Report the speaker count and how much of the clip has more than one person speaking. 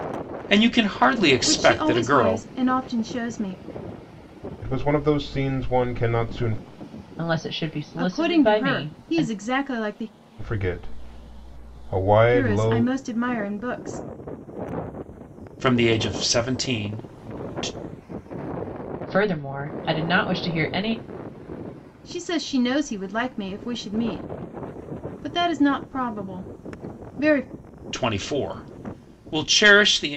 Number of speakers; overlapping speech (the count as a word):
four, about 10%